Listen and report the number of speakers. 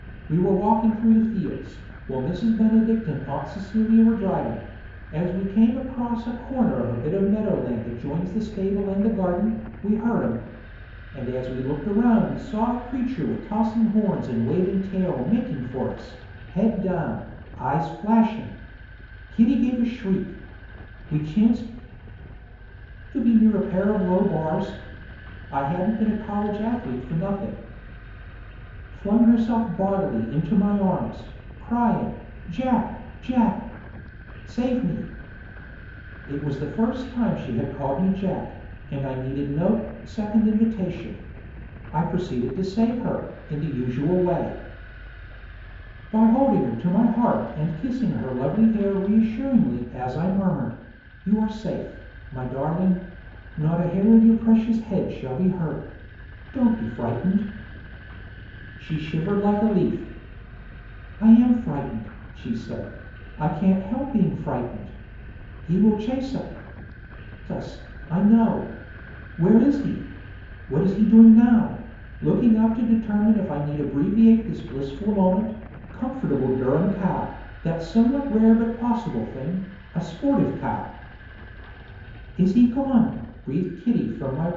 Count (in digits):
1